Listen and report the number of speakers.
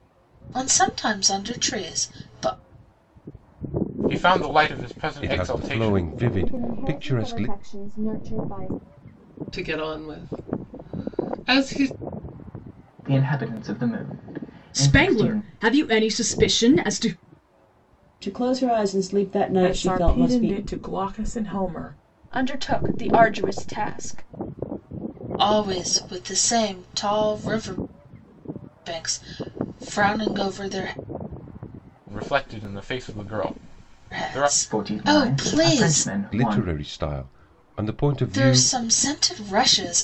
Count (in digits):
10